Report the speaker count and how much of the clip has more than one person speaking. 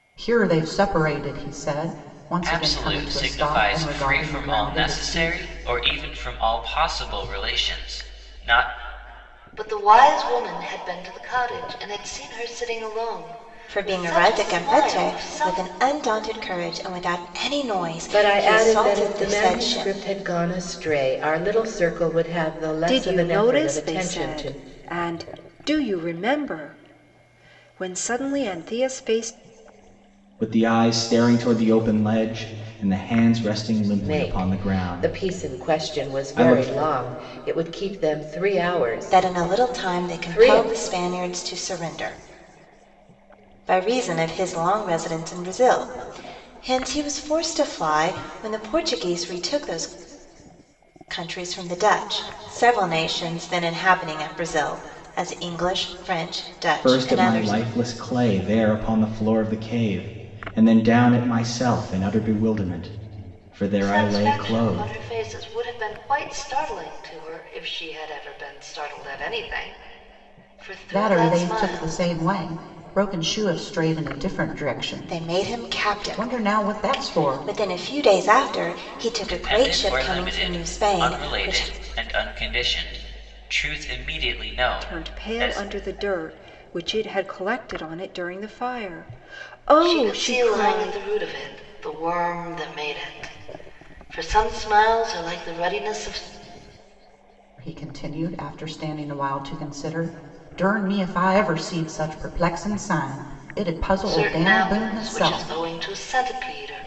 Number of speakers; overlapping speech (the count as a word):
seven, about 23%